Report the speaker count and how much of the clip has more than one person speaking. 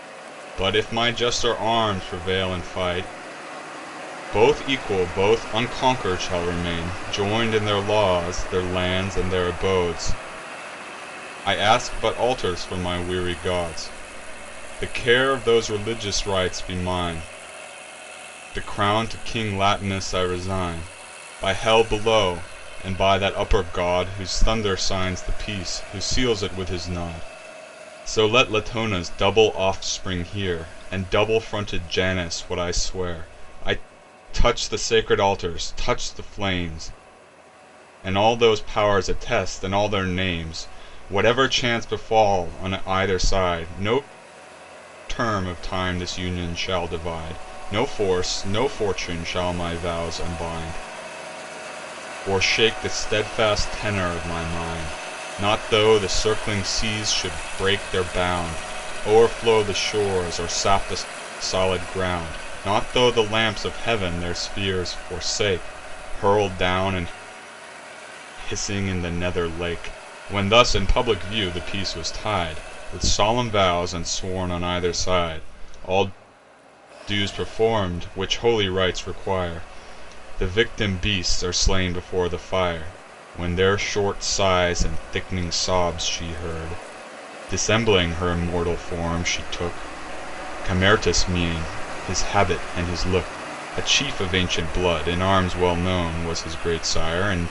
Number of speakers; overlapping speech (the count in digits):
1, no overlap